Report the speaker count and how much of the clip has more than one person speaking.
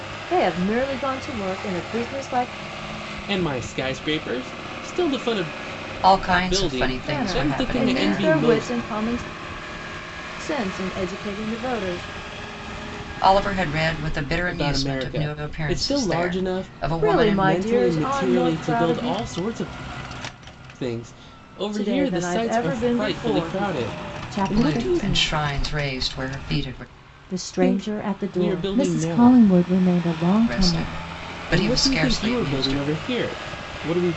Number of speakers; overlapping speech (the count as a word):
three, about 41%